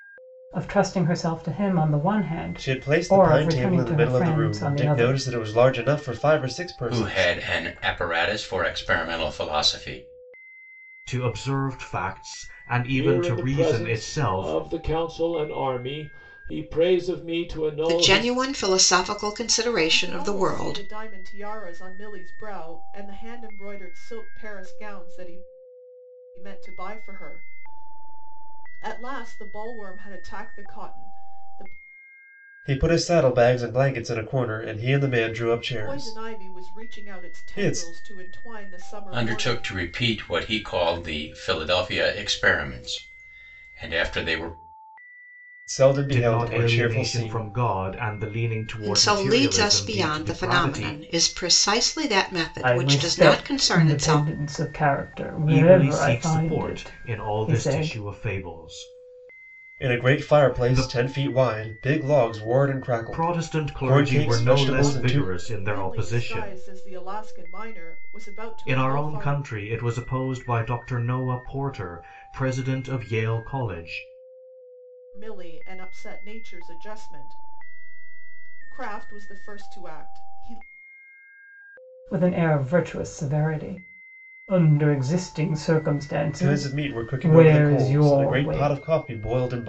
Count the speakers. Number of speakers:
seven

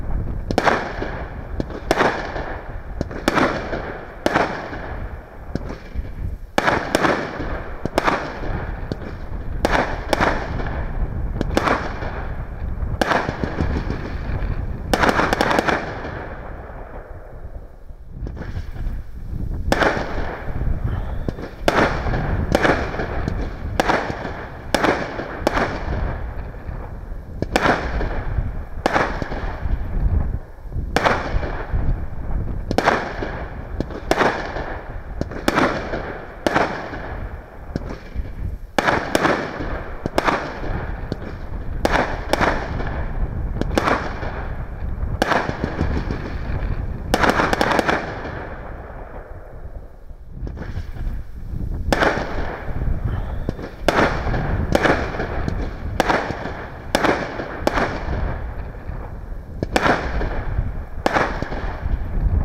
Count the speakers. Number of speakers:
zero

